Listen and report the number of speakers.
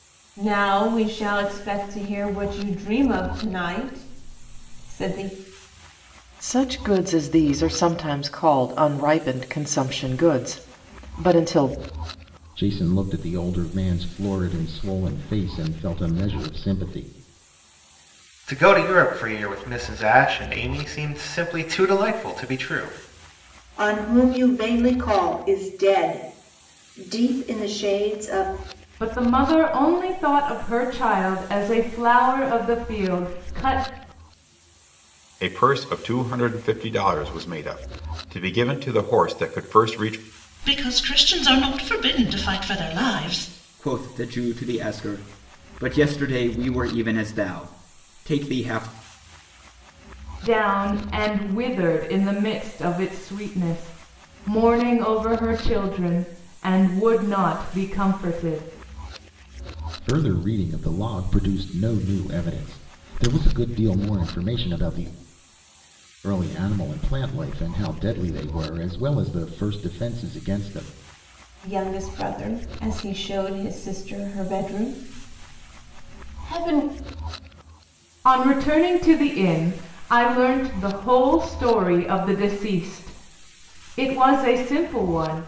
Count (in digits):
9